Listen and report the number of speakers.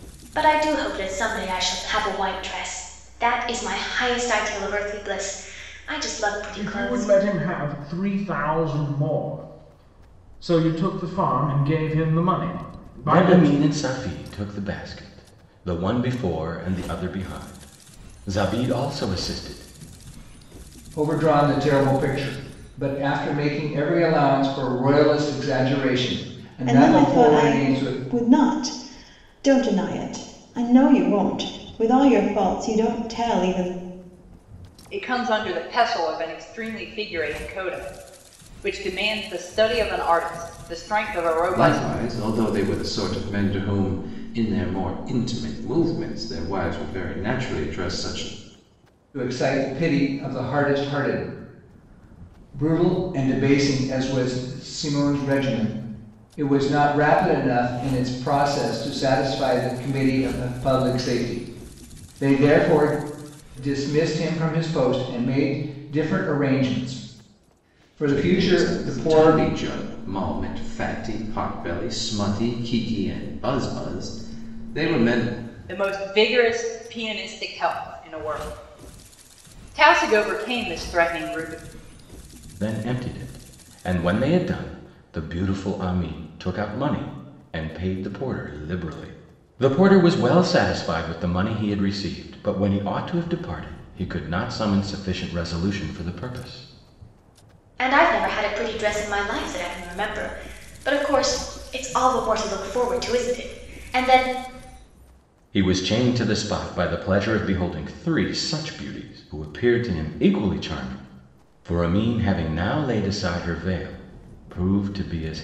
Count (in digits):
7